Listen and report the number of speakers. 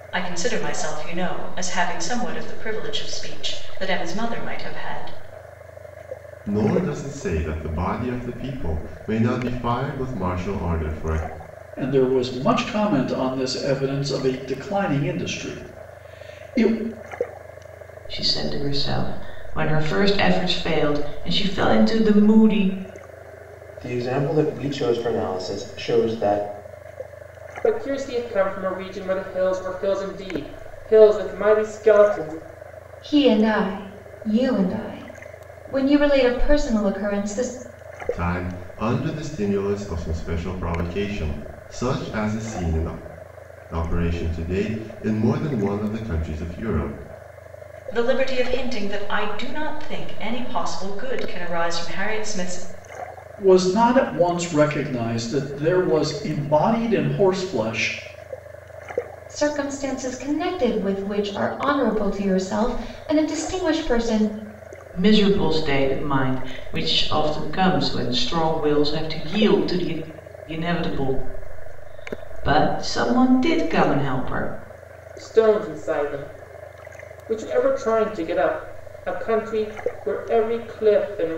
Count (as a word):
seven